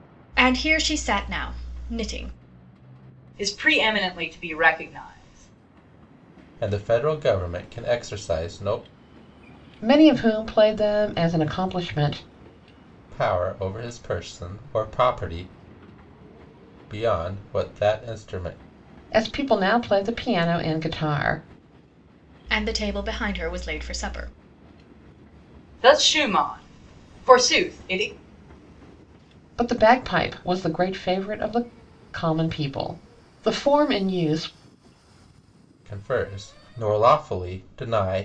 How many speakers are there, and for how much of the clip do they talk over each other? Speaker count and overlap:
4, no overlap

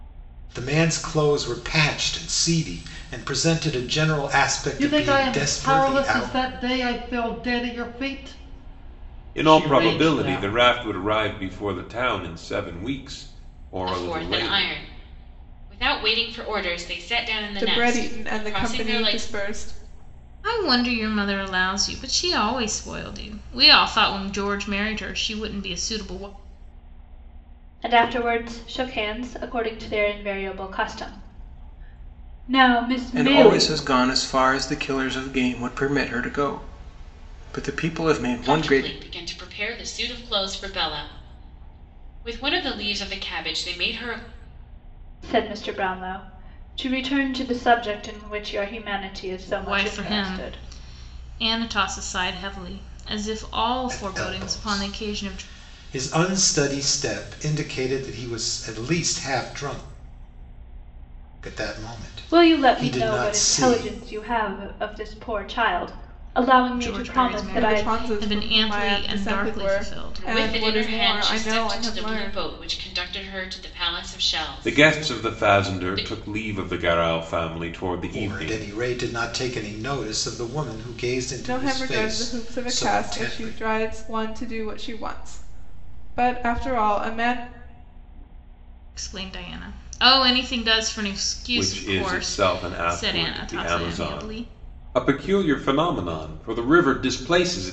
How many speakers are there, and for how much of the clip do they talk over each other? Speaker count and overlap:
8, about 25%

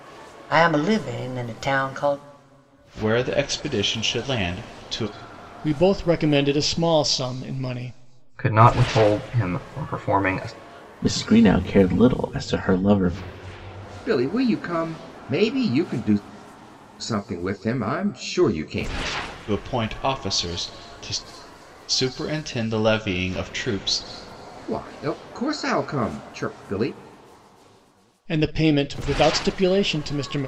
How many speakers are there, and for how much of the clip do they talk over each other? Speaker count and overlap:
6, no overlap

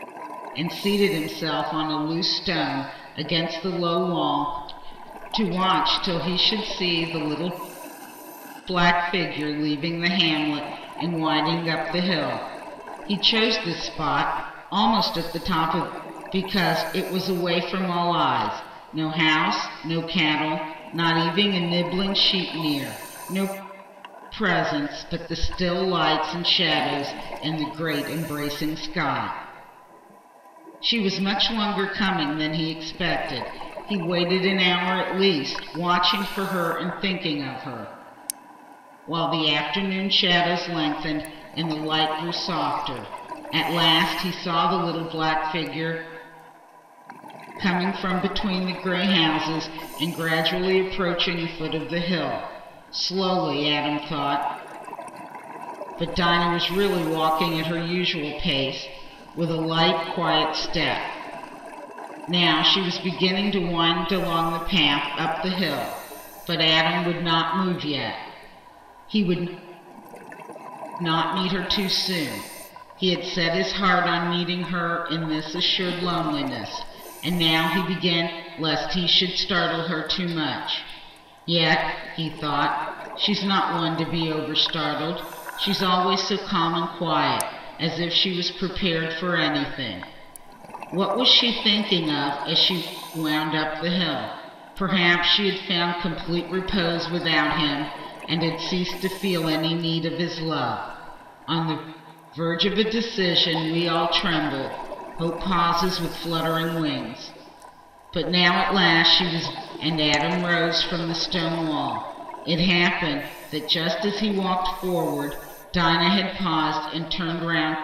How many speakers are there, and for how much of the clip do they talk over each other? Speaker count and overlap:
1, no overlap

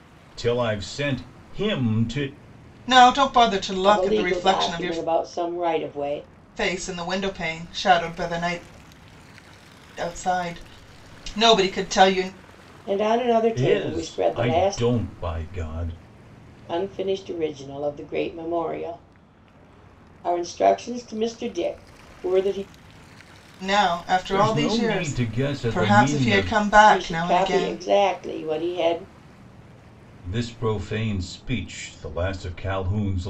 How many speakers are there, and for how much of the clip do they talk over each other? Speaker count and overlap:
3, about 16%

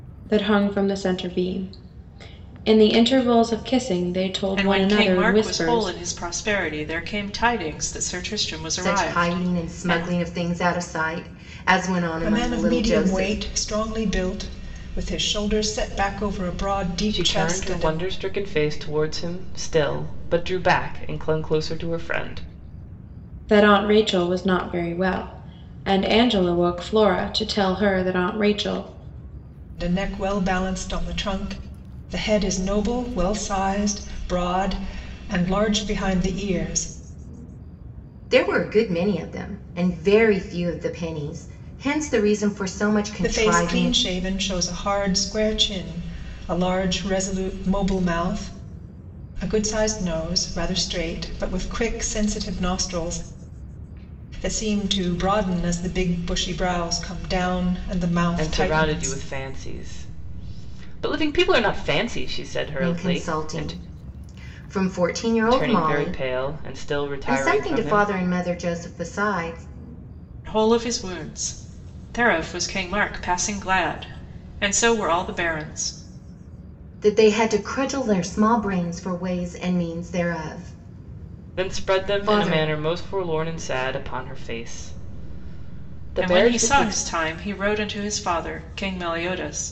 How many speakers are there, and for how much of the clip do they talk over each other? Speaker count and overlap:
5, about 13%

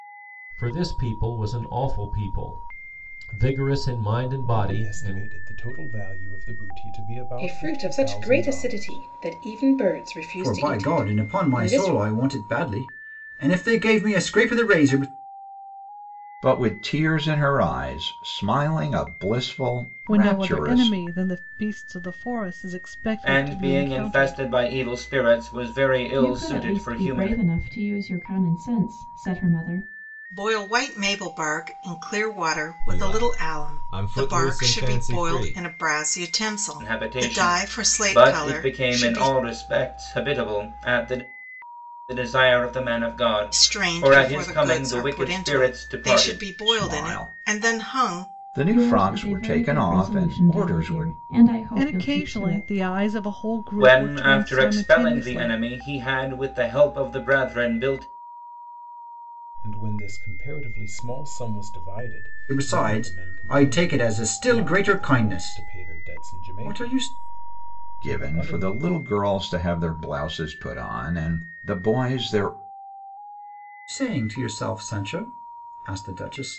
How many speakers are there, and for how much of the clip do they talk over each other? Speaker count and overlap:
10, about 37%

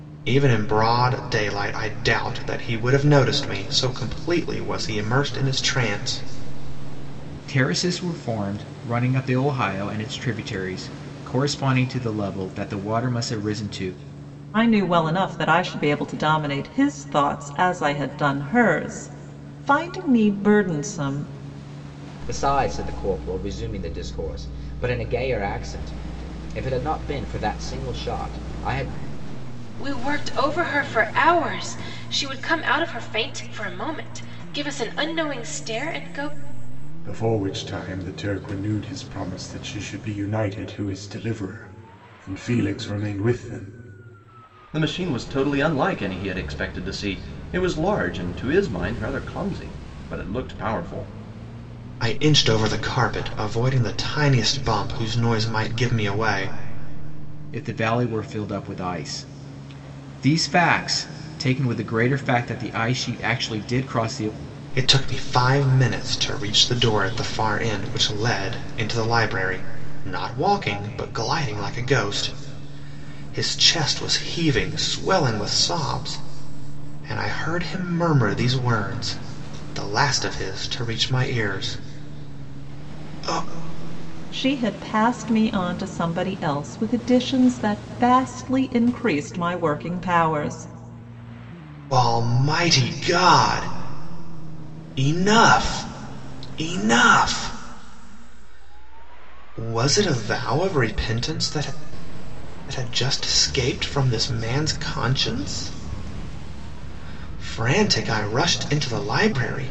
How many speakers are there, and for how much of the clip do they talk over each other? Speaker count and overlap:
7, no overlap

